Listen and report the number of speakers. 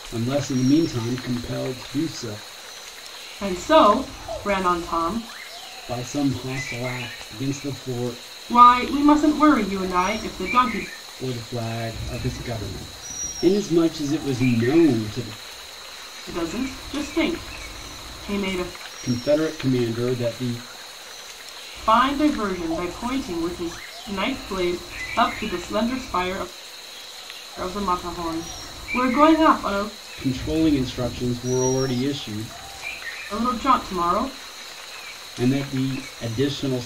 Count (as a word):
two